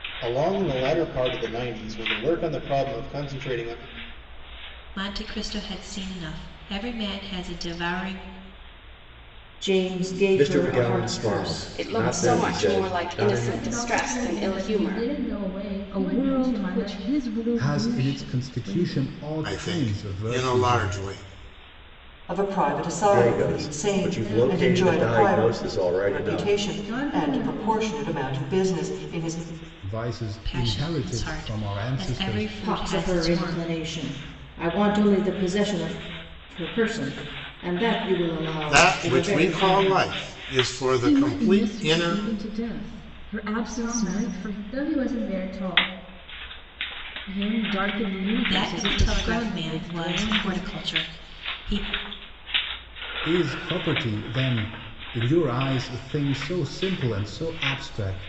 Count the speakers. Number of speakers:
ten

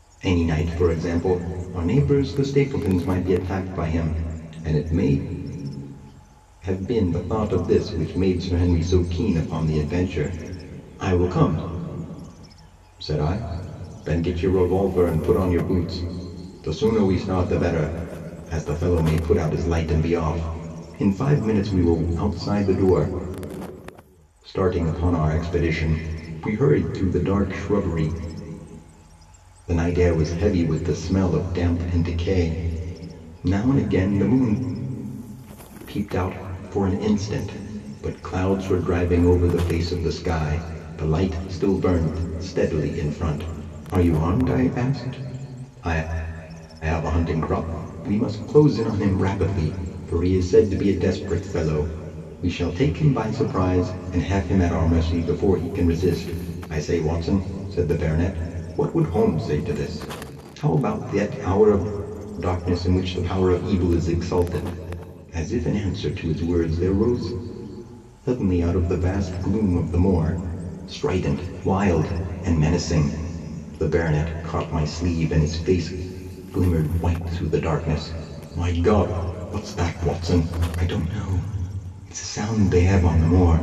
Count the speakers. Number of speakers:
one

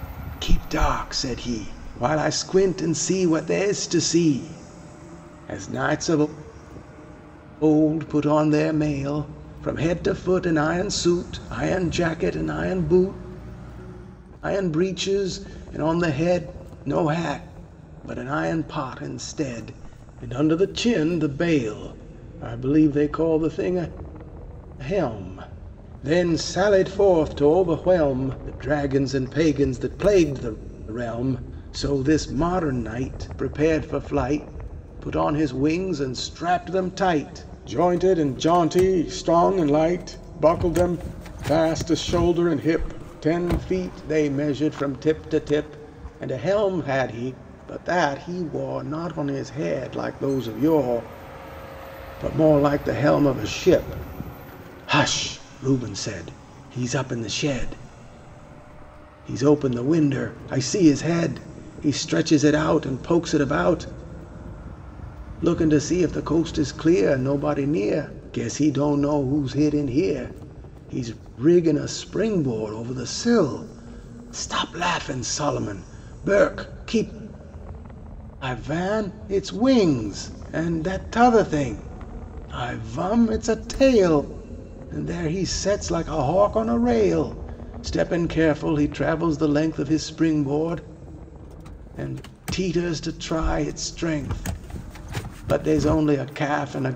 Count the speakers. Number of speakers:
one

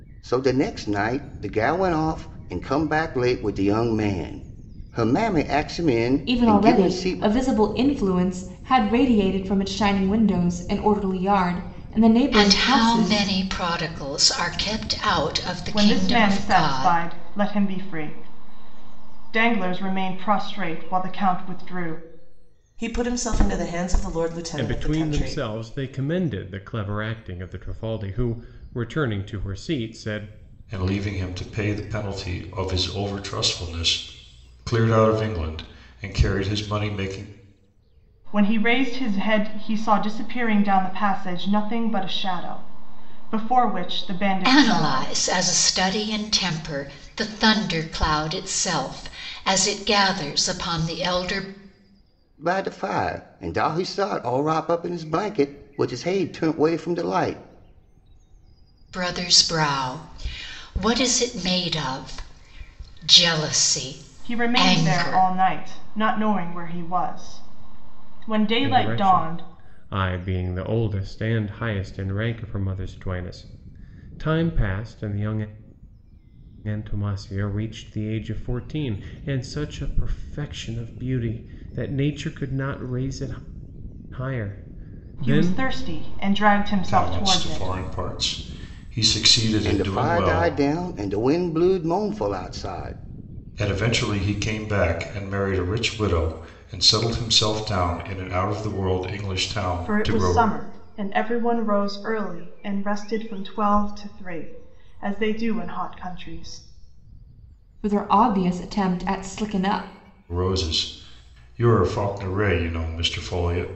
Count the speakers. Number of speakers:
seven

